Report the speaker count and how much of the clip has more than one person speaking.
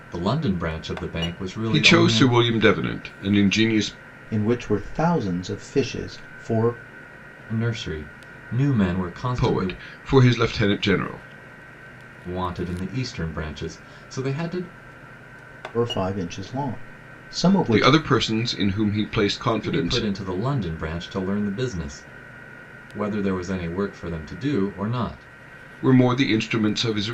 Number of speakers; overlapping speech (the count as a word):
three, about 7%